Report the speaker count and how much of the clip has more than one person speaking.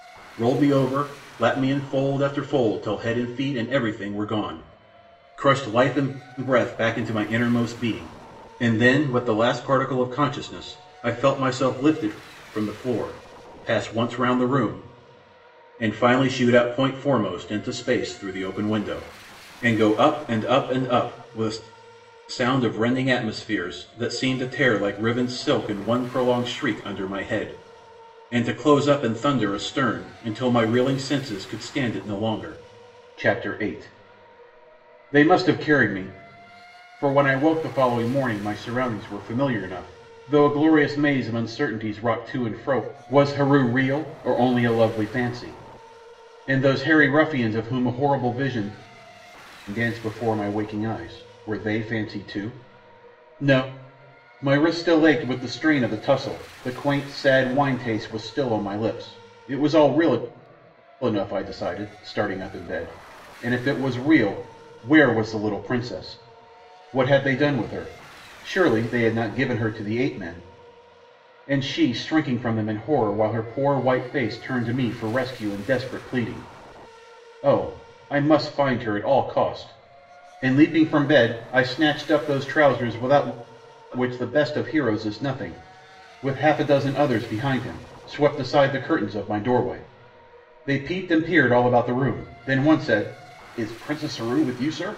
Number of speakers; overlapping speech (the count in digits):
1, no overlap